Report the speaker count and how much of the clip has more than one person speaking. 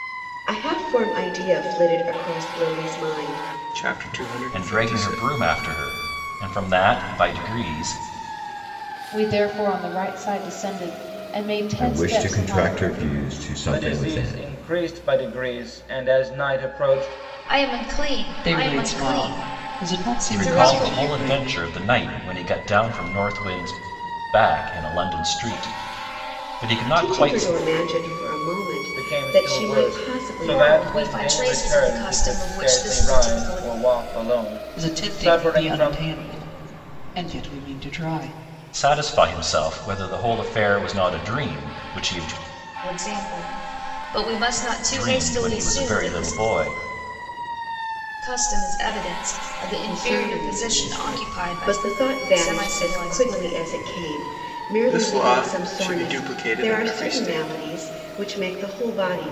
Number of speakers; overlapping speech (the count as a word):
eight, about 34%